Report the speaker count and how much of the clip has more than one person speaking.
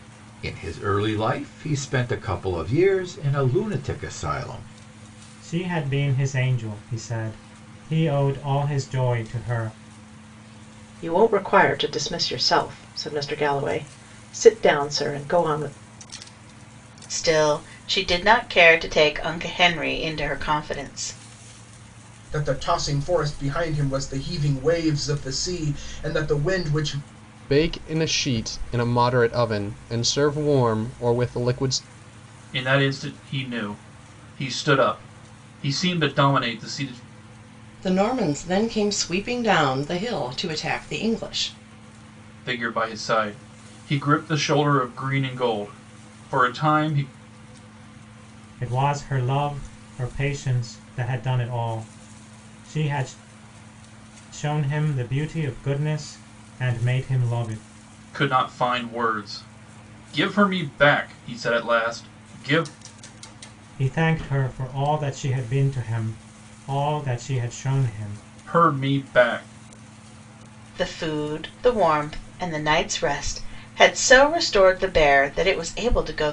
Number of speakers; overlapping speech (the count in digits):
8, no overlap